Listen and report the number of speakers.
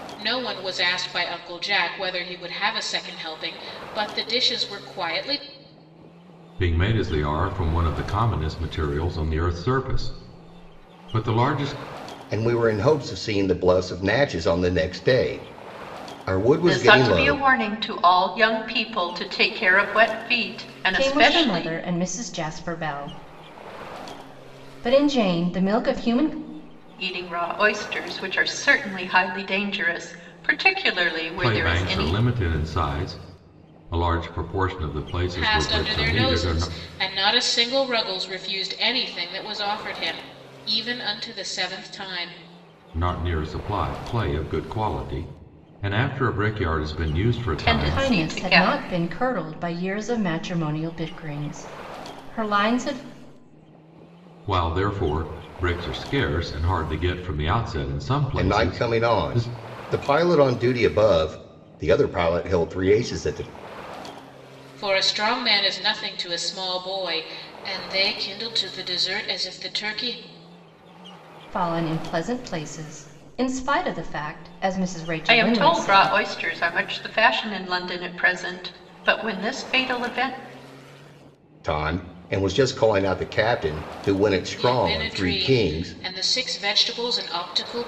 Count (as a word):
five